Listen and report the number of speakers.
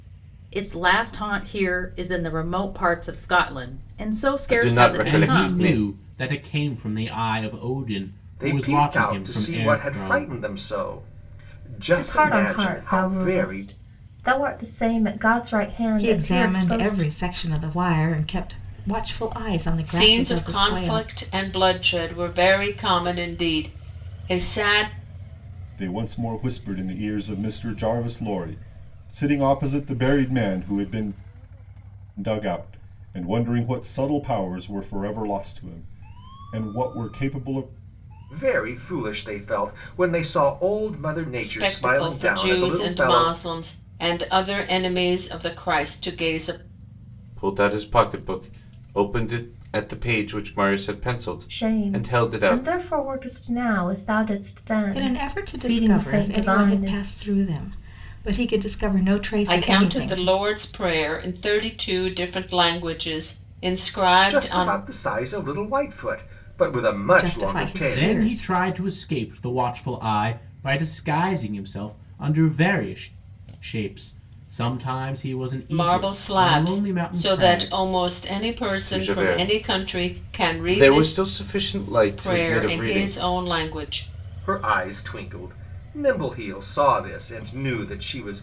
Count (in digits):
8